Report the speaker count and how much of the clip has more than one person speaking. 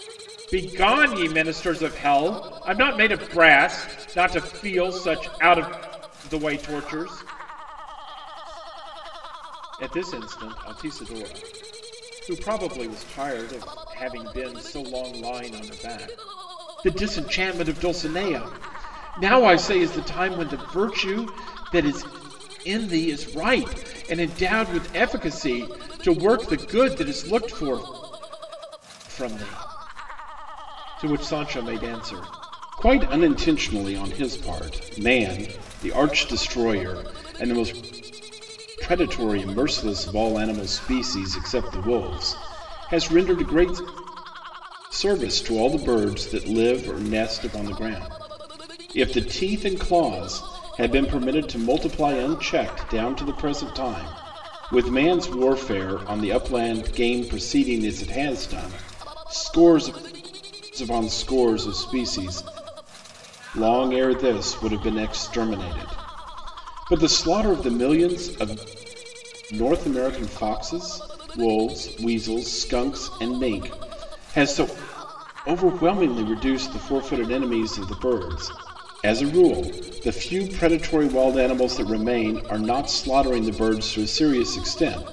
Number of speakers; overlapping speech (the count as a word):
one, no overlap